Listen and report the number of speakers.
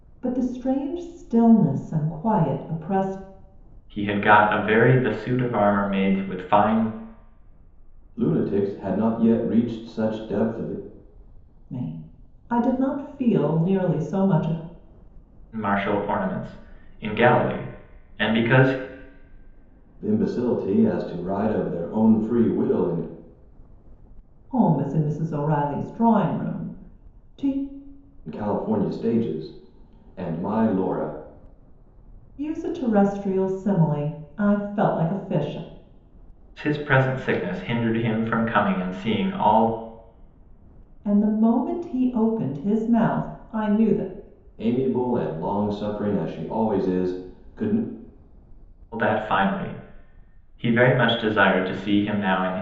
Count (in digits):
3